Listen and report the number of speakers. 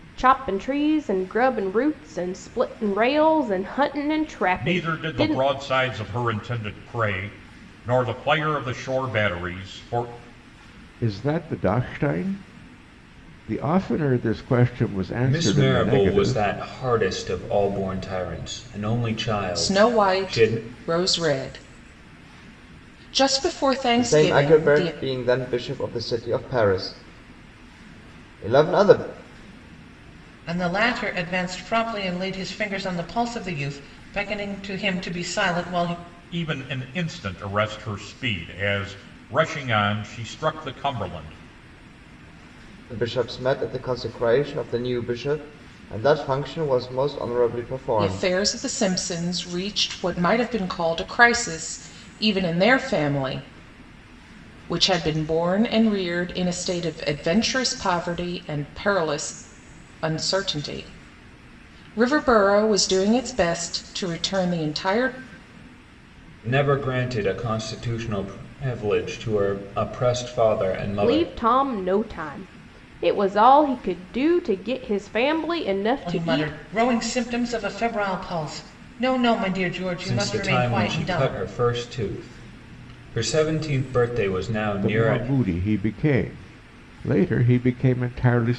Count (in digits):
7